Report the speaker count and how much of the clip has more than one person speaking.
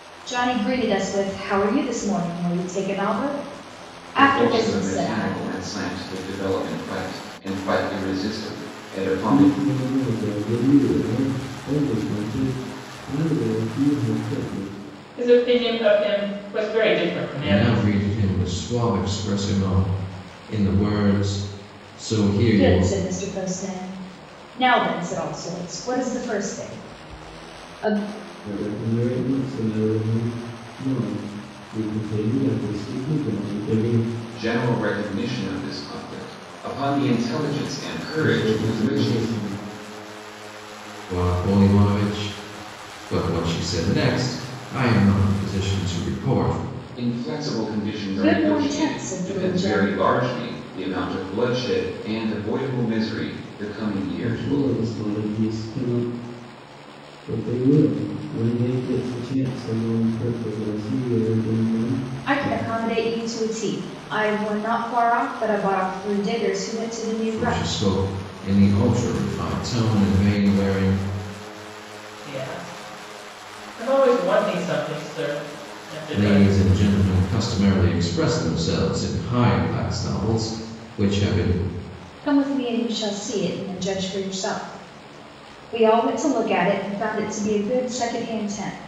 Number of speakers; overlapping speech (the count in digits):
5, about 8%